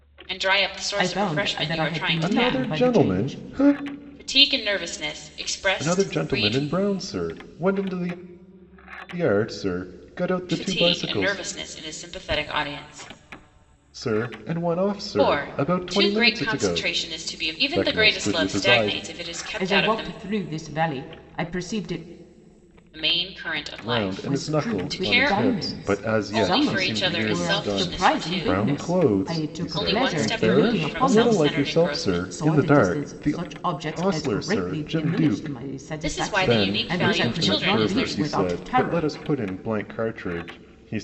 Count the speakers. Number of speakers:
3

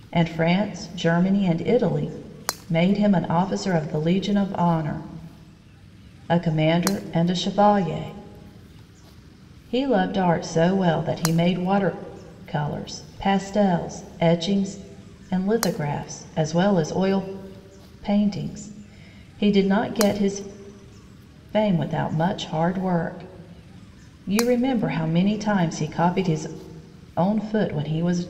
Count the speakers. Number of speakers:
1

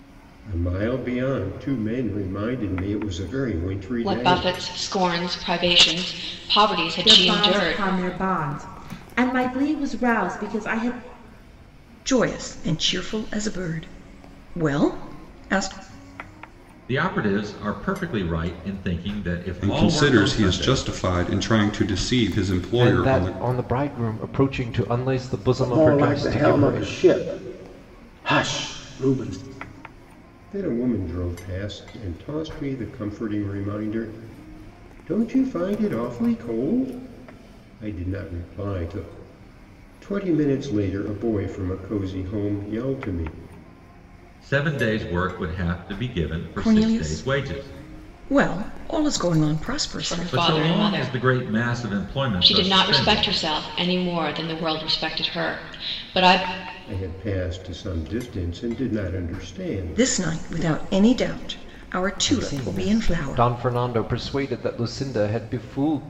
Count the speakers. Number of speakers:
8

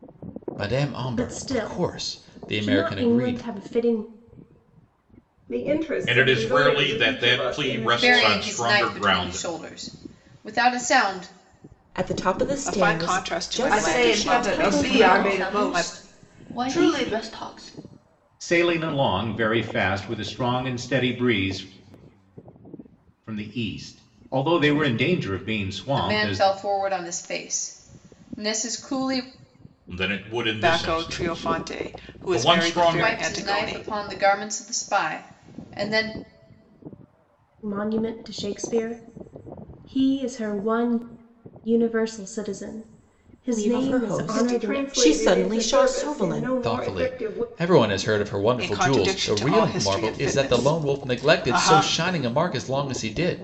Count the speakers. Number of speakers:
10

